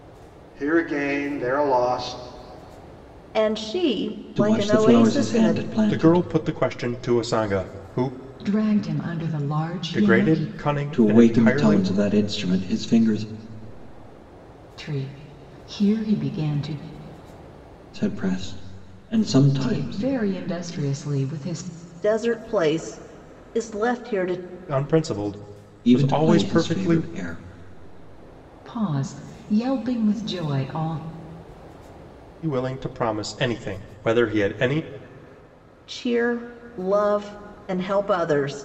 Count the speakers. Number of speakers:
five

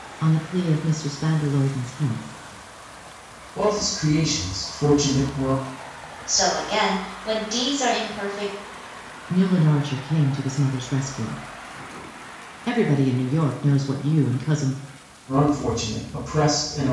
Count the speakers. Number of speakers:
three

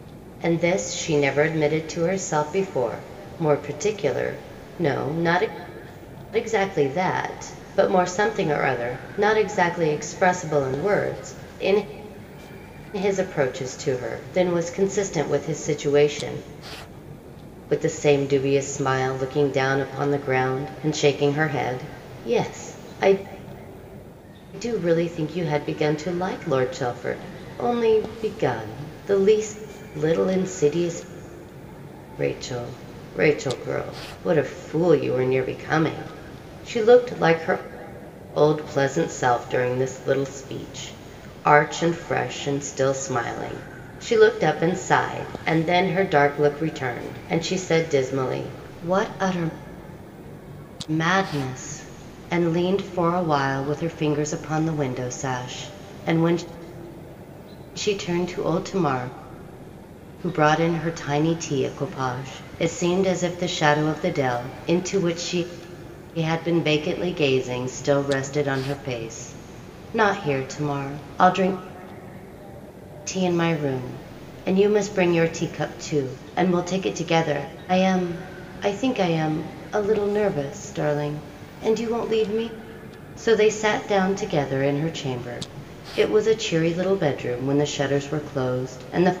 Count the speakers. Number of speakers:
one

